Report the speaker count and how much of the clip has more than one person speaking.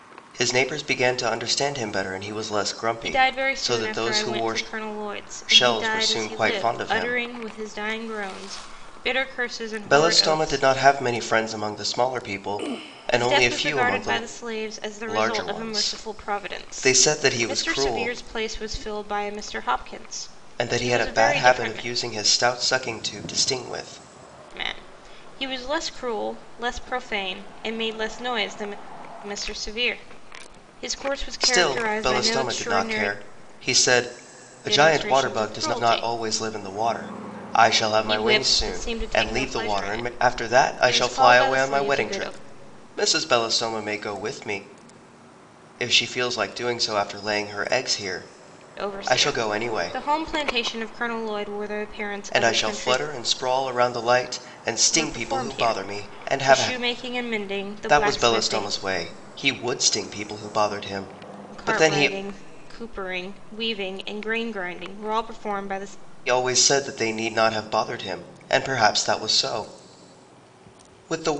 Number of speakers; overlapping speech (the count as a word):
two, about 31%